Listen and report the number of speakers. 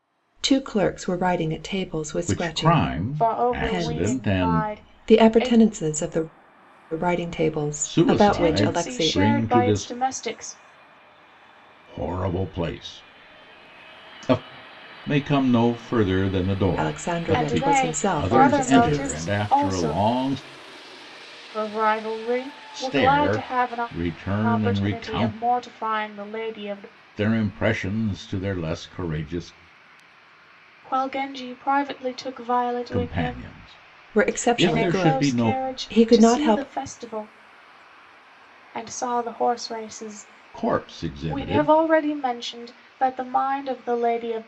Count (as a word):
three